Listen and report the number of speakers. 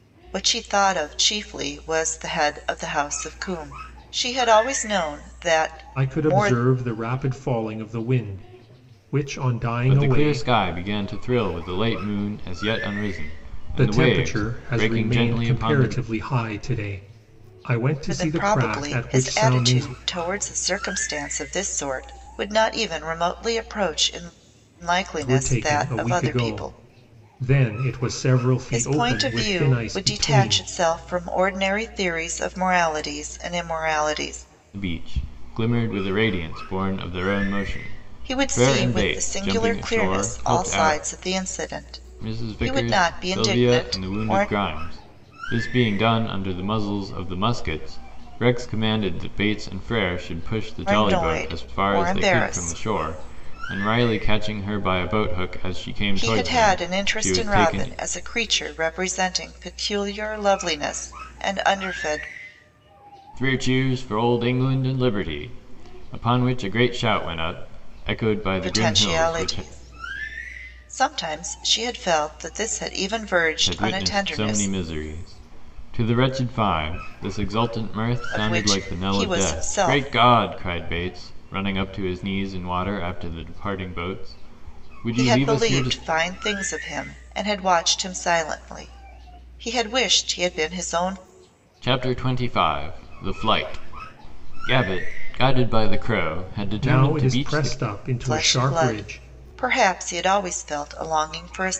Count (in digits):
3